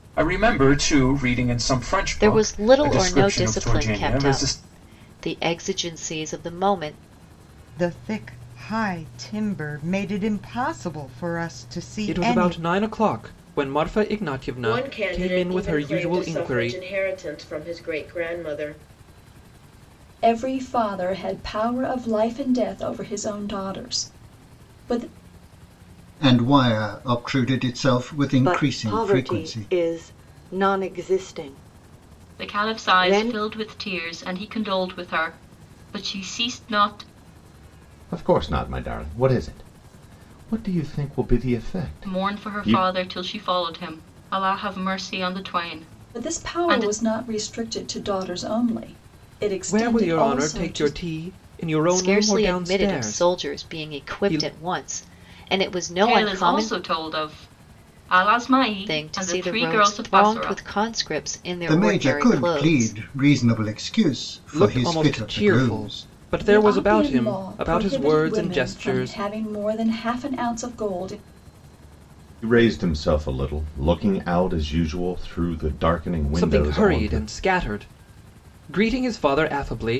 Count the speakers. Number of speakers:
ten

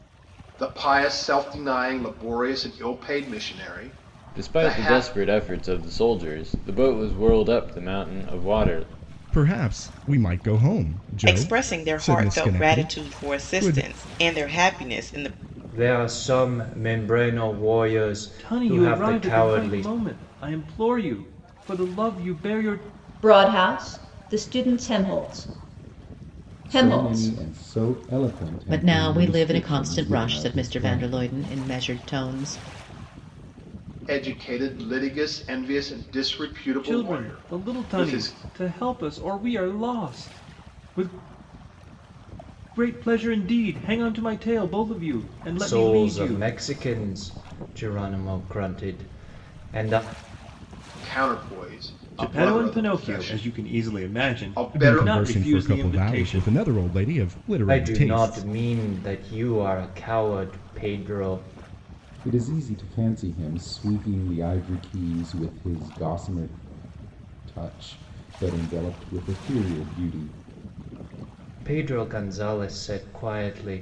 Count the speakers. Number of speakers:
nine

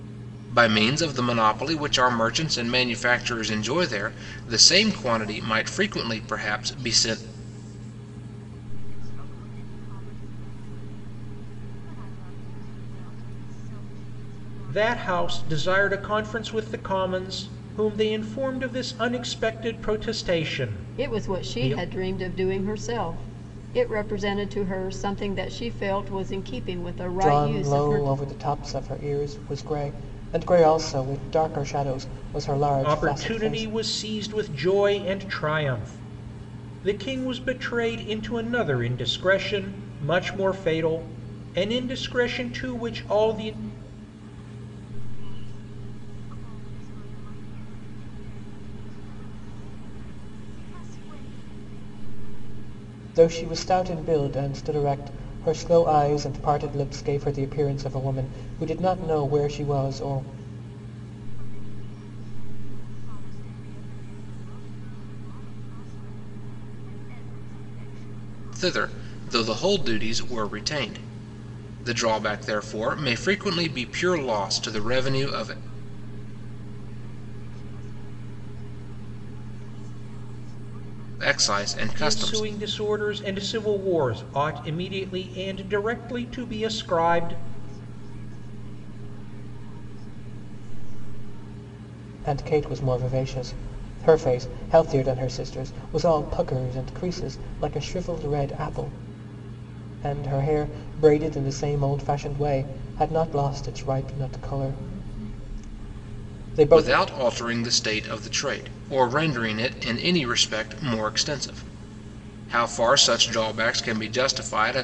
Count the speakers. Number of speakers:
five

